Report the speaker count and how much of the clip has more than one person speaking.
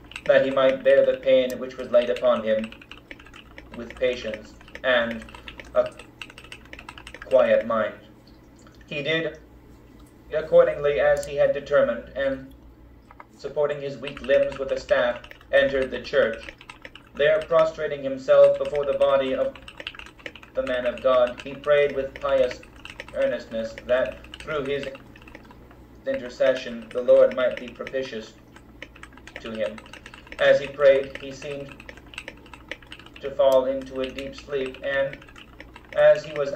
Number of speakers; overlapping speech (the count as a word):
one, no overlap